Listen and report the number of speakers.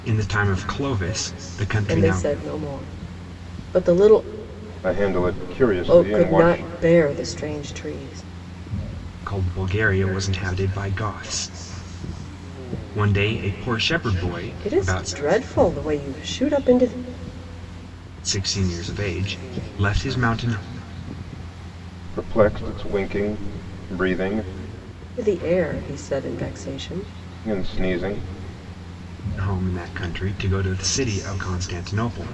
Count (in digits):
3